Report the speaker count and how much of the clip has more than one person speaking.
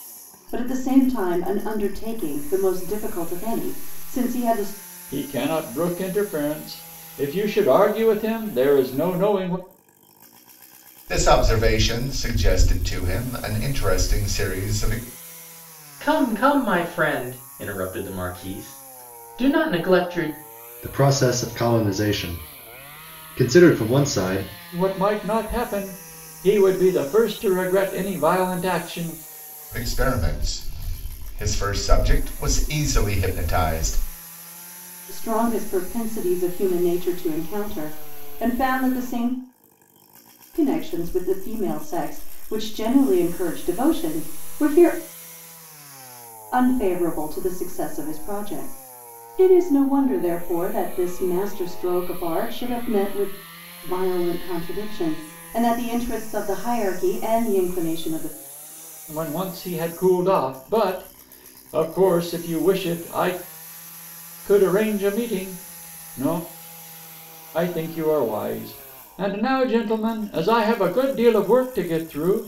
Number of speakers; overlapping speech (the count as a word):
five, no overlap